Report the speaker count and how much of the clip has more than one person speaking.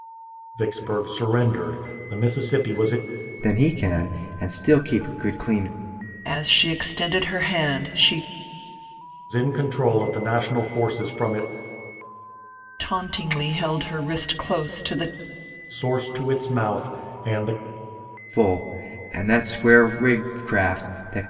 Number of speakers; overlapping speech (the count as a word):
three, no overlap